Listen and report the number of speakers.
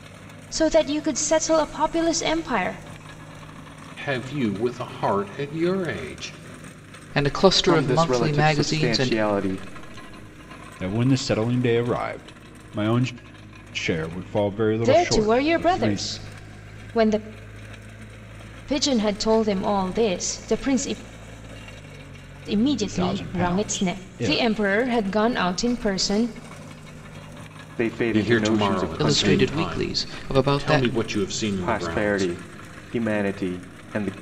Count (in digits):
5